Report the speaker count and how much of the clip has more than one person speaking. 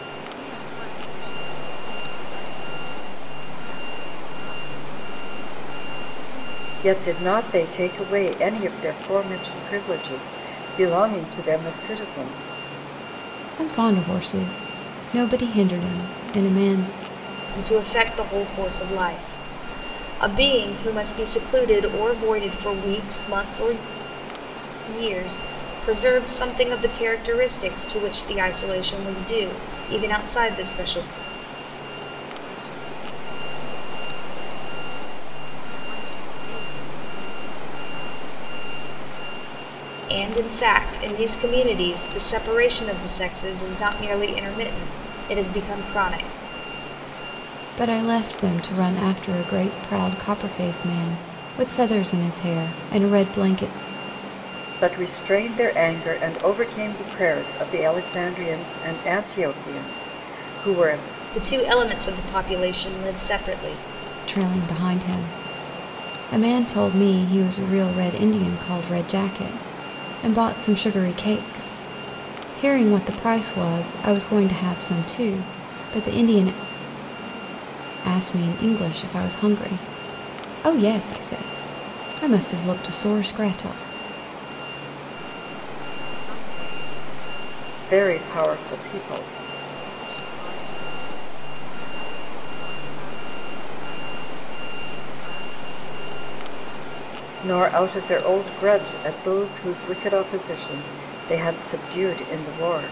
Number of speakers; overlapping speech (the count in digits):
4, no overlap